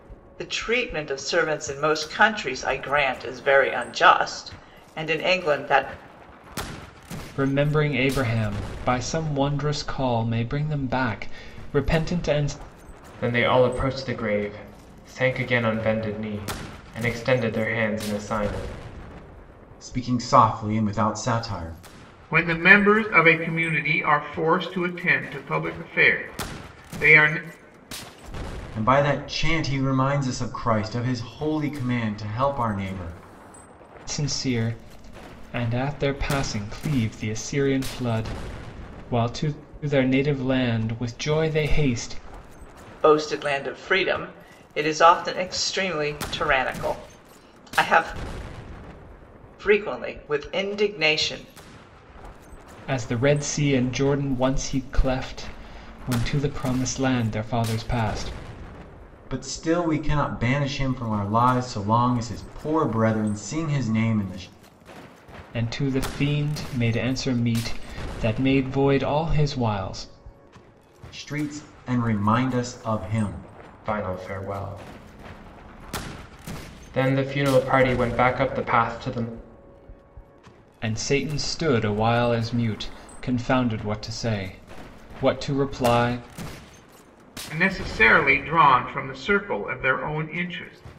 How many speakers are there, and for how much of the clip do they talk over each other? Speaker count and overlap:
5, no overlap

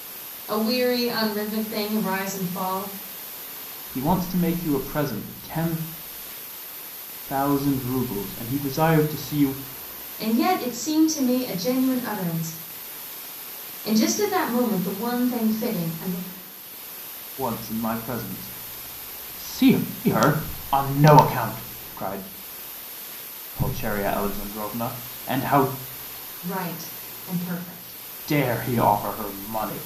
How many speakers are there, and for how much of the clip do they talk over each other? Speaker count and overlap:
2, no overlap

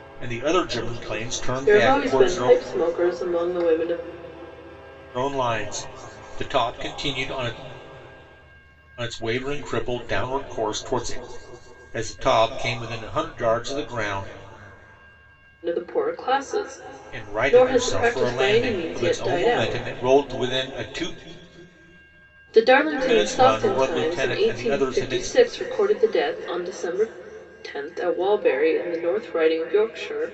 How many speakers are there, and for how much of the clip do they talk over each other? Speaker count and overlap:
2, about 19%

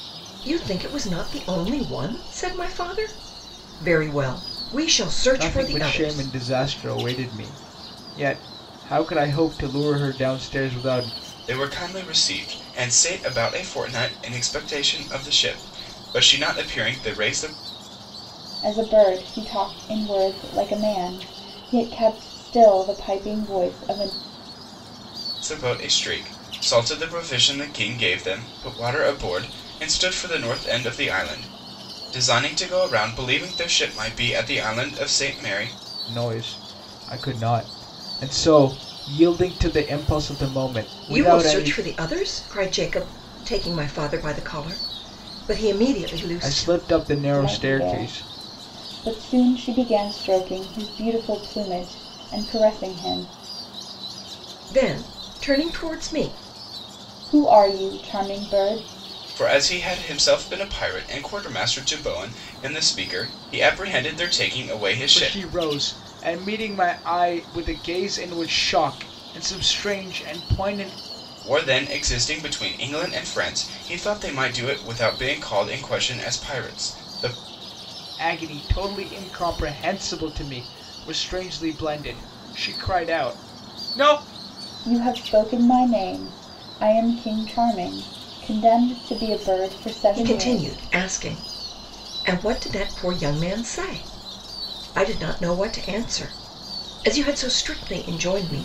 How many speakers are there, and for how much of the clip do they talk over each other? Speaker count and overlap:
4, about 4%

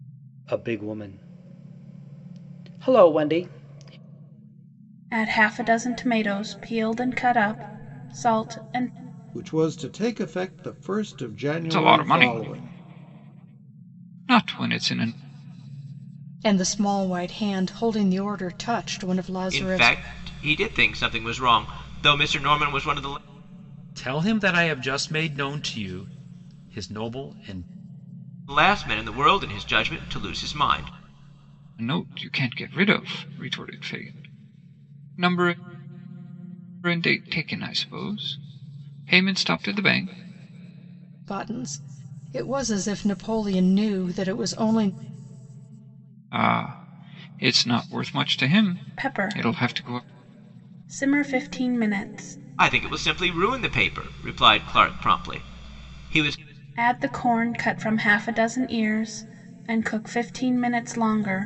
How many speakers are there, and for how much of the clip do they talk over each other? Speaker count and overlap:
7, about 5%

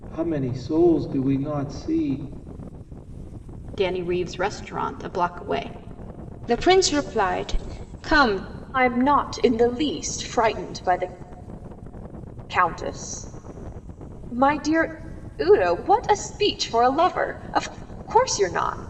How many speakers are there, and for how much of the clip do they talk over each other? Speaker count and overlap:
4, no overlap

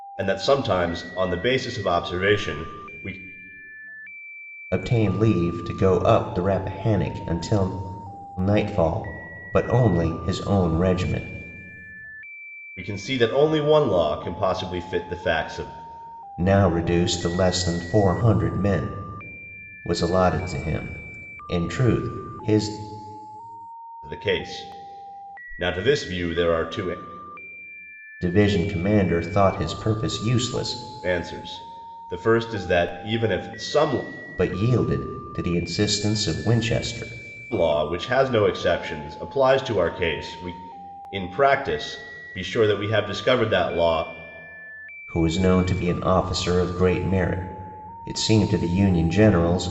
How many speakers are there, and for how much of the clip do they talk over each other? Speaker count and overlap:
2, no overlap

